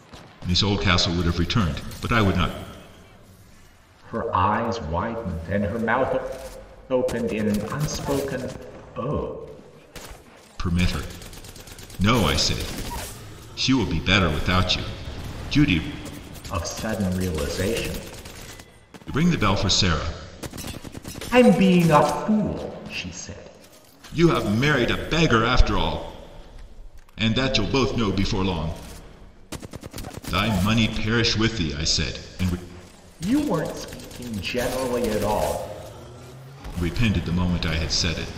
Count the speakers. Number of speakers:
two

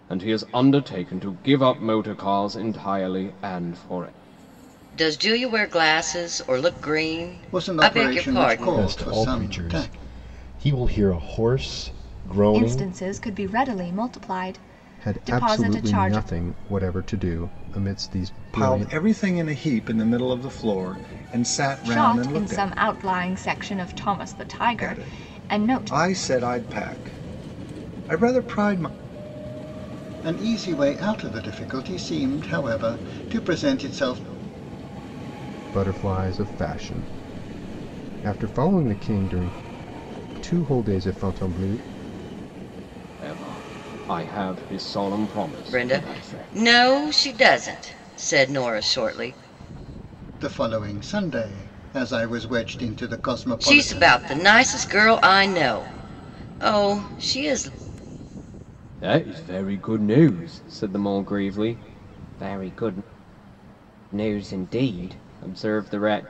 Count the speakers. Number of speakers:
seven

